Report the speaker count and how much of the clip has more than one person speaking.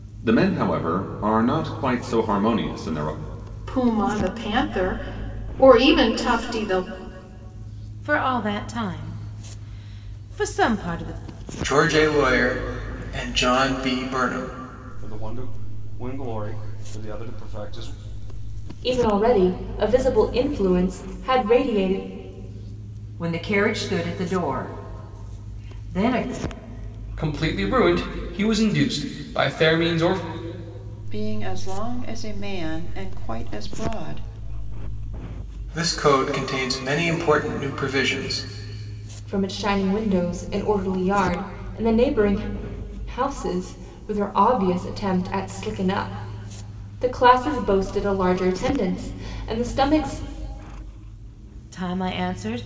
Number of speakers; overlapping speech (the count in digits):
9, no overlap